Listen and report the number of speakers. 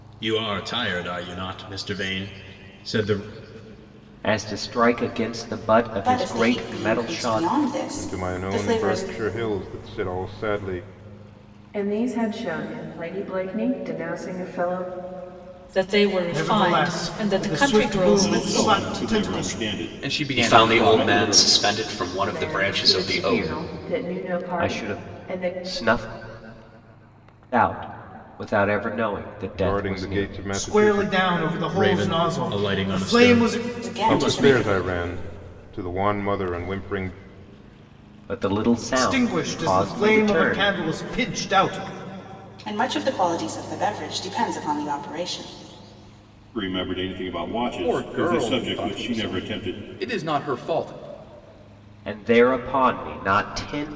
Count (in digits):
10